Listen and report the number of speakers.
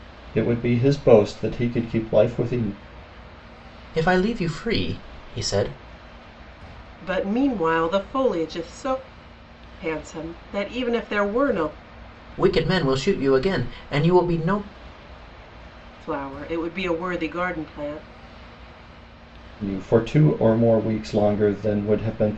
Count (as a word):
three